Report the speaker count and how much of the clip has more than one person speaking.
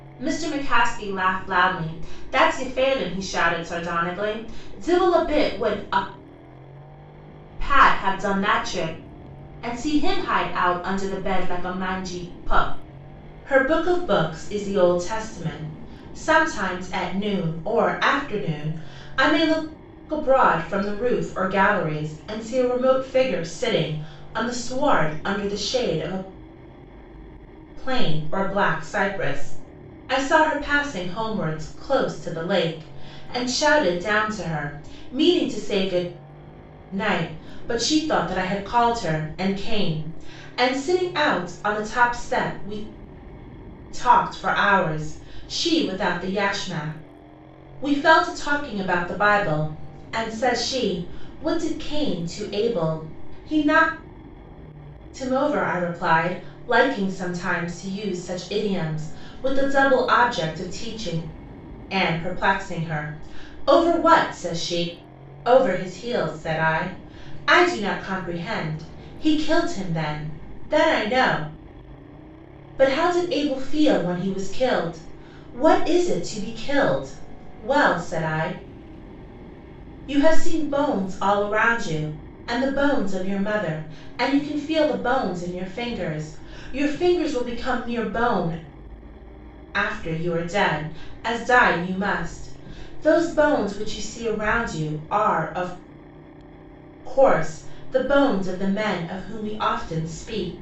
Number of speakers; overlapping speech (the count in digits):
1, no overlap